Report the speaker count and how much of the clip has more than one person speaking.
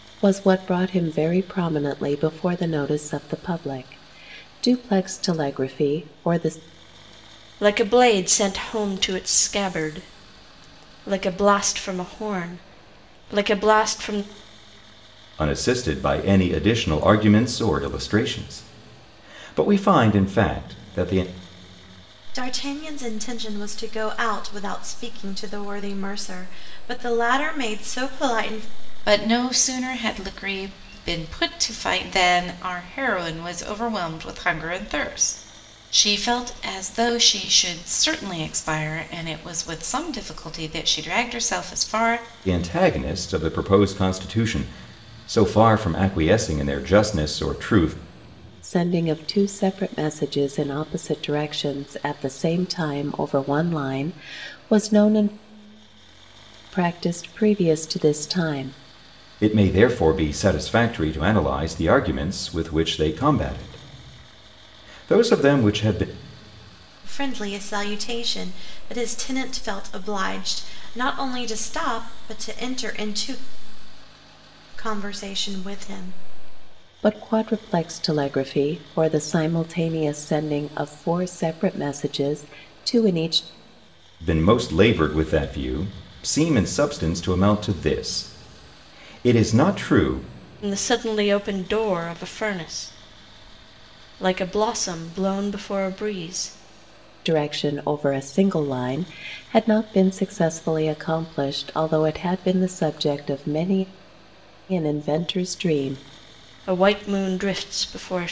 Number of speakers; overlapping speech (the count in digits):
5, no overlap